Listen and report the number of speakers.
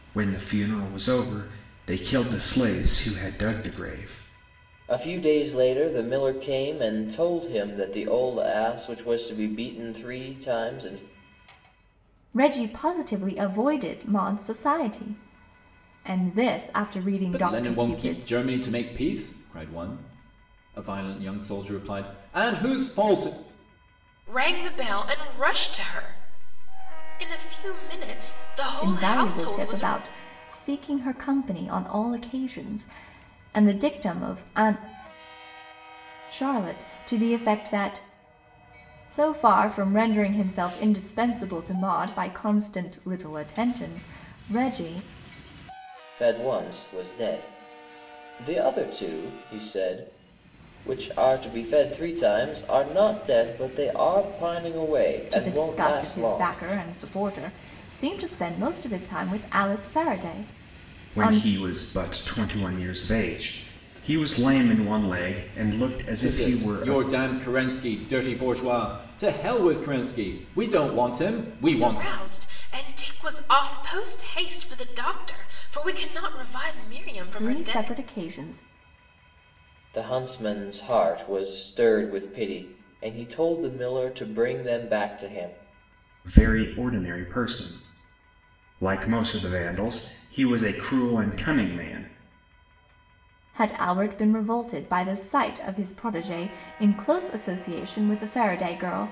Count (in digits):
5